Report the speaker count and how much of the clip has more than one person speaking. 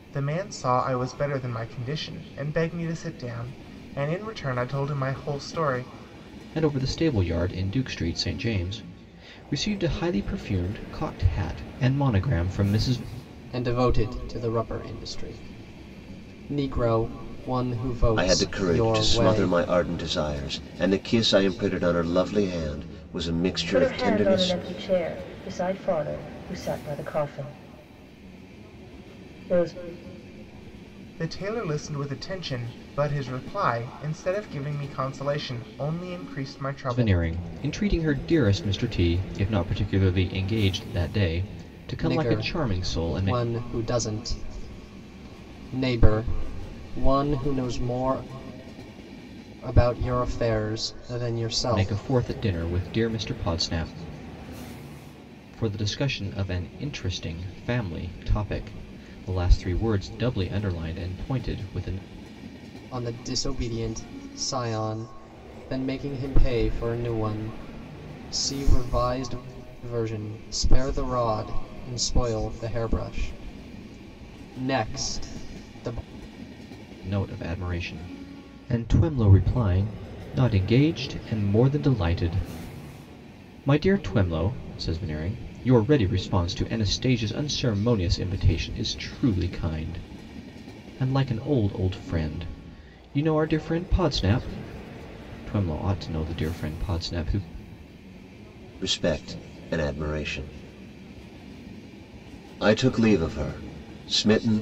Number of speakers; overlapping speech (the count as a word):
five, about 4%